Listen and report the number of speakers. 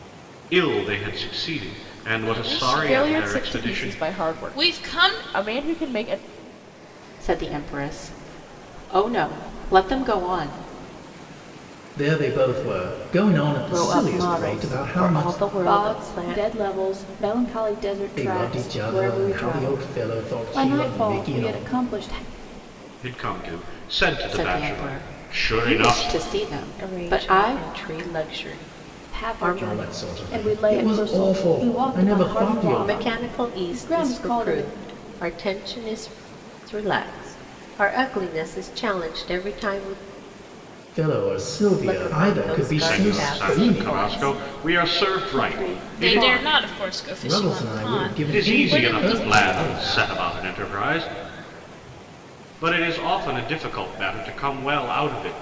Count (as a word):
seven